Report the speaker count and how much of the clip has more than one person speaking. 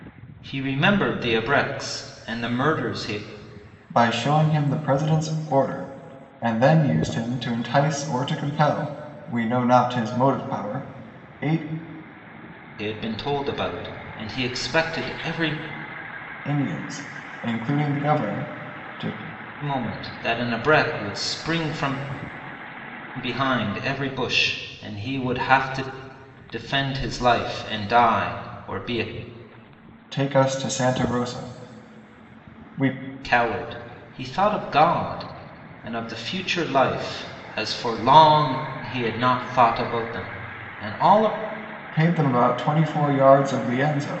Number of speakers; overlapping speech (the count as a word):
two, no overlap